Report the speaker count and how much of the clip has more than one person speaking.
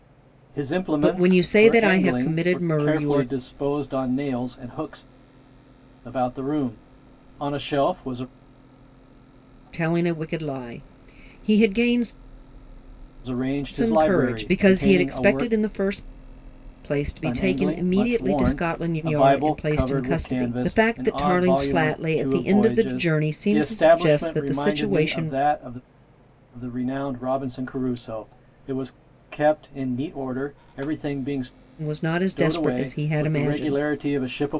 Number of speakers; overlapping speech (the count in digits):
2, about 40%